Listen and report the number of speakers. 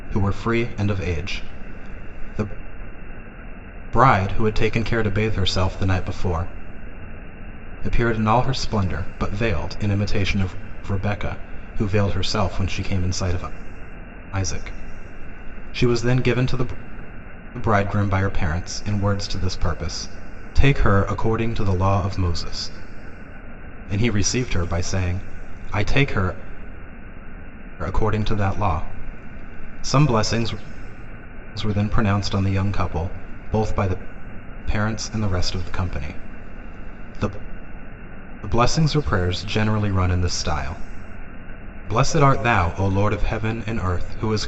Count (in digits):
1